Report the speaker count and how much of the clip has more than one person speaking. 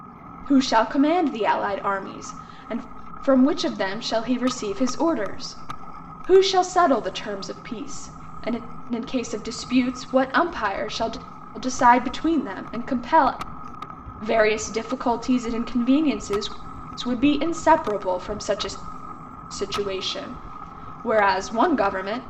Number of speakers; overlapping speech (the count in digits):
1, no overlap